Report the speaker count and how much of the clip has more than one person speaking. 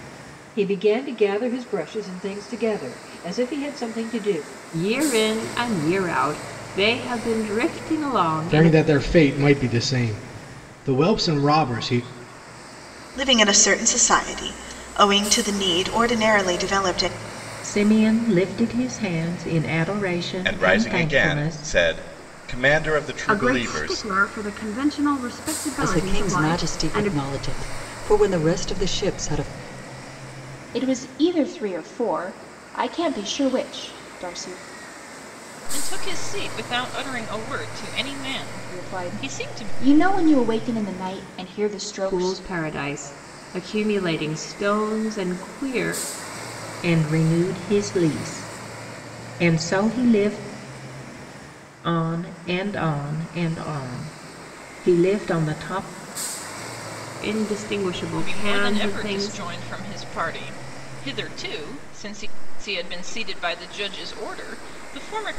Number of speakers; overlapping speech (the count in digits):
10, about 10%